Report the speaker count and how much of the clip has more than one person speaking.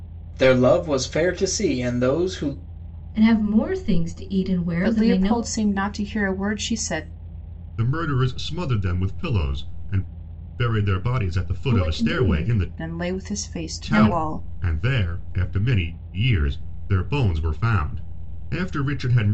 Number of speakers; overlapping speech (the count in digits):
4, about 18%